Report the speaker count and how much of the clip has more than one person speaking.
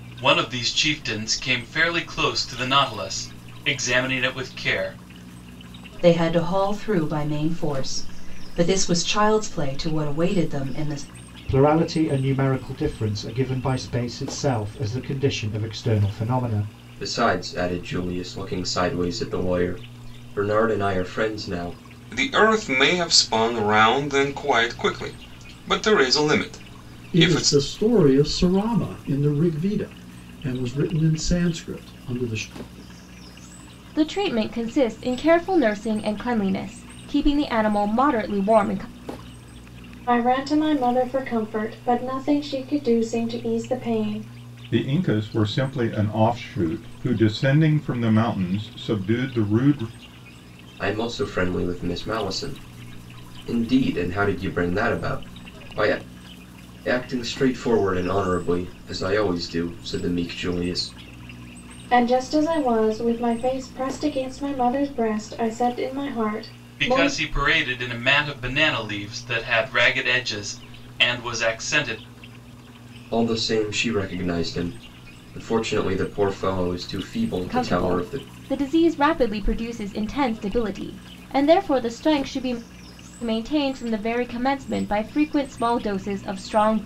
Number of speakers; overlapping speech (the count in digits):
9, about 2%